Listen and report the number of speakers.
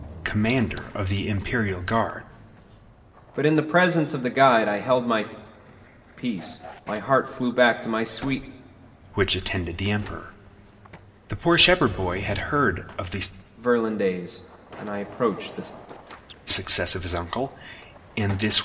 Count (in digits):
2